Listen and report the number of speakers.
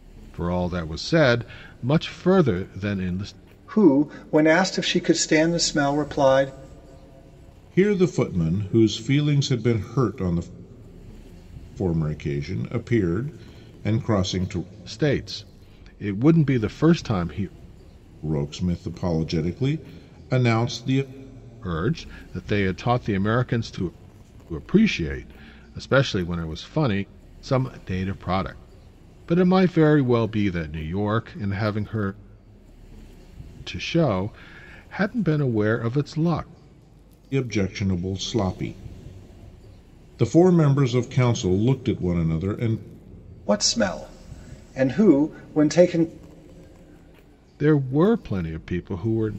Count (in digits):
3